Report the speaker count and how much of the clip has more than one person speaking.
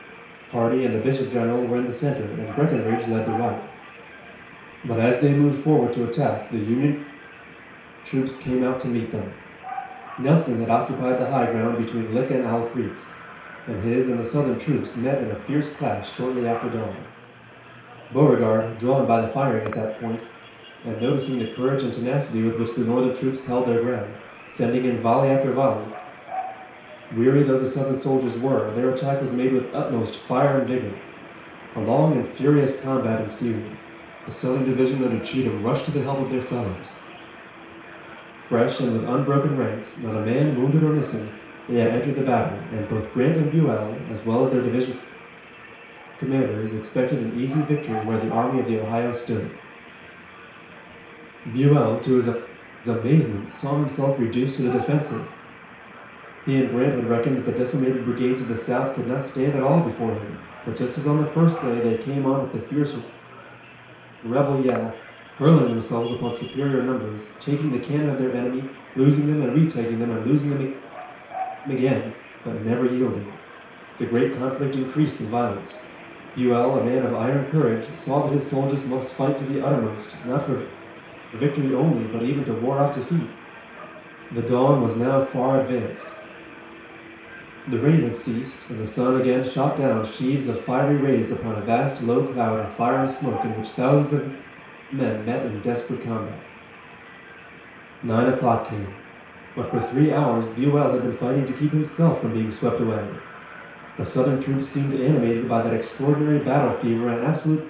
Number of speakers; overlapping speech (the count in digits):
1, no overlap